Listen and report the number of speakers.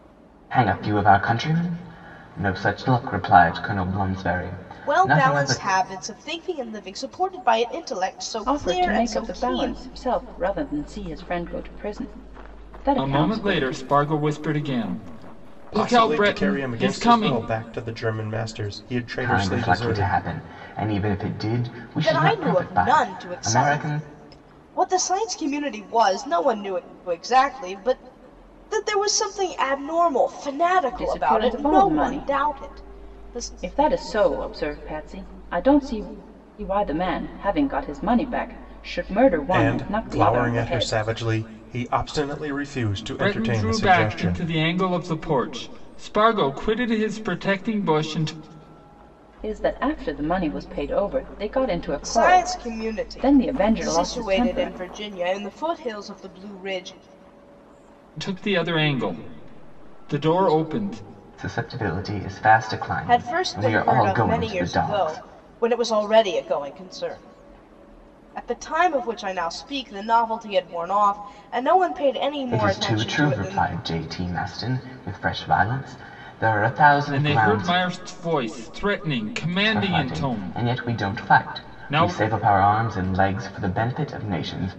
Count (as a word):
five